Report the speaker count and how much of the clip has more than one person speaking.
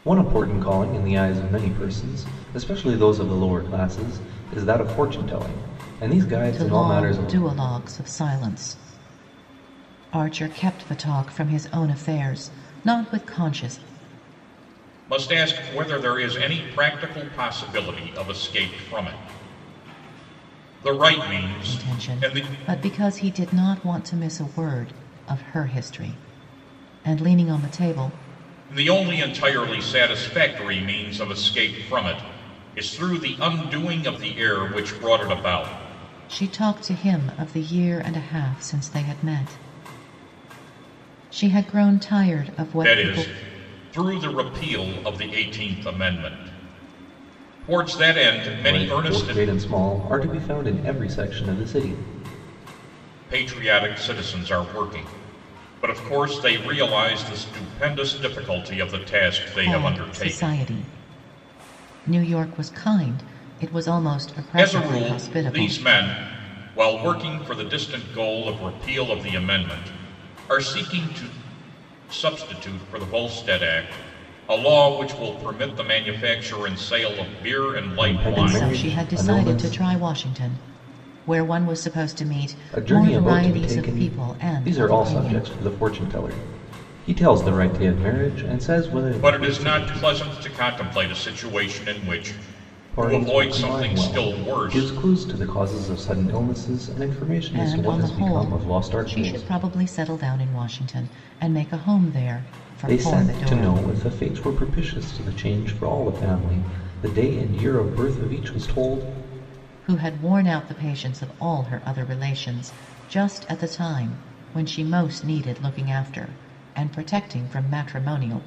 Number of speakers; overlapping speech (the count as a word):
three, about 14%